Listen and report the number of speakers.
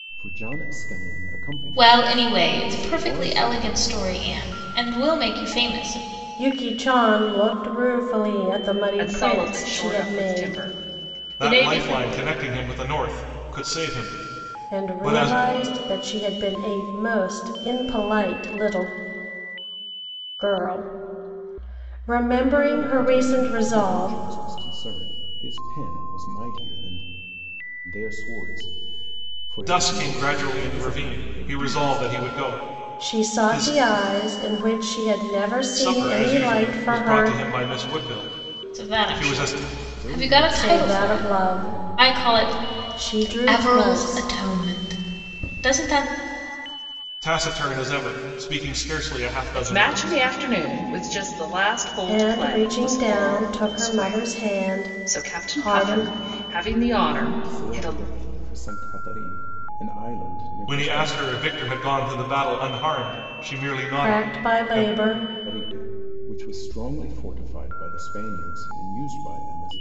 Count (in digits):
5